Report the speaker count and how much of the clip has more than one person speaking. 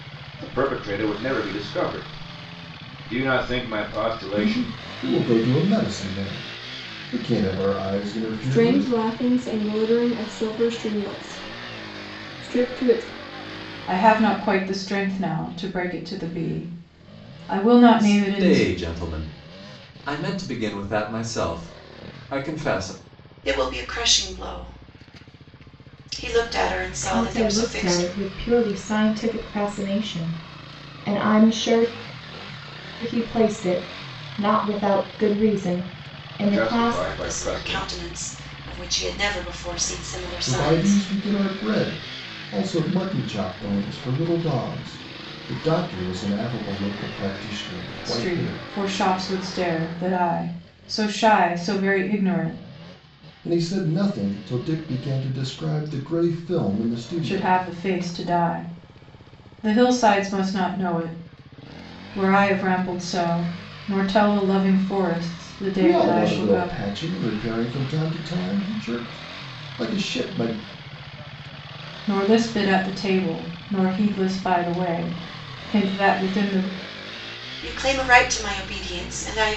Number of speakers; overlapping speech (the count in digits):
7, about 9%